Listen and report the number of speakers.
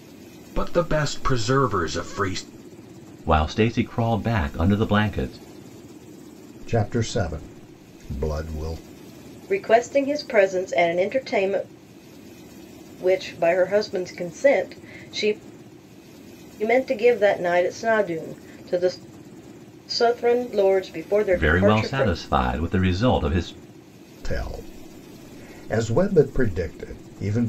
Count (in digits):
4